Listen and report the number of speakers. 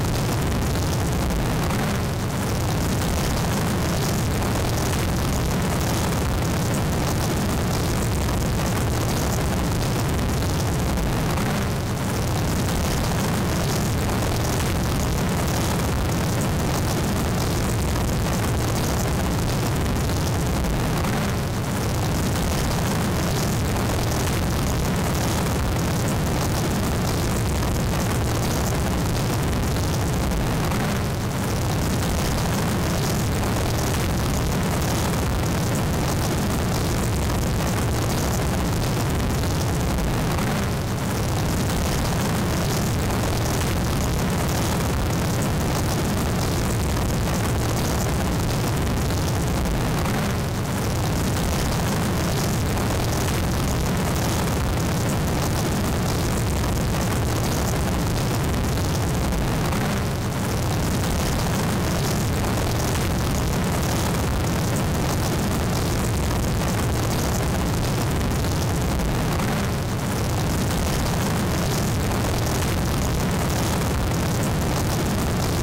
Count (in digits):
0